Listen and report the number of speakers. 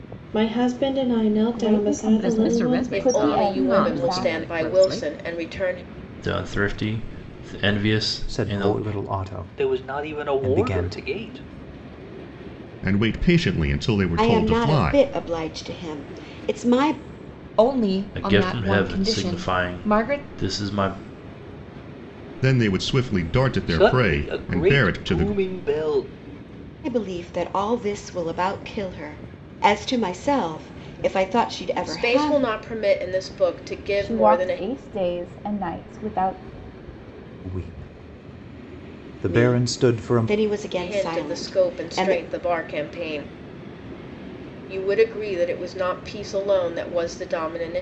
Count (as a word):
ten